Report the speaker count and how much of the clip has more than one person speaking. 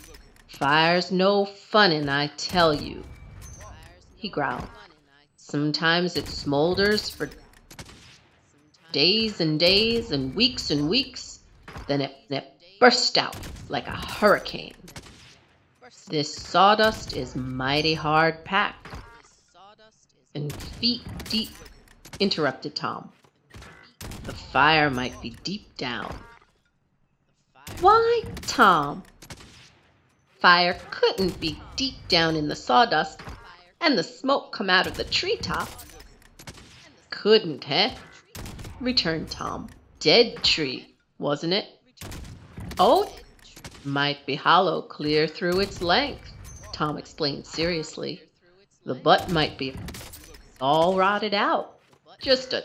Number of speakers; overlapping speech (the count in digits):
1, no overlap